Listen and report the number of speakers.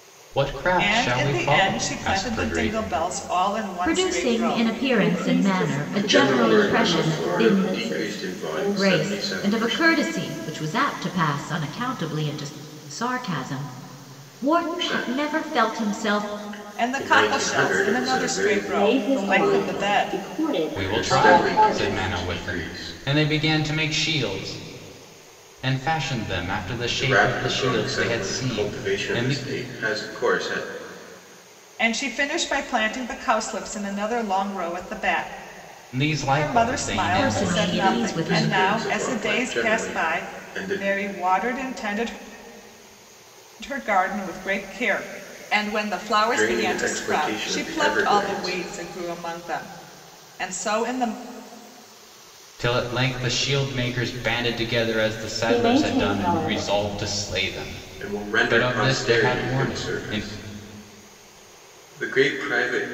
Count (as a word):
five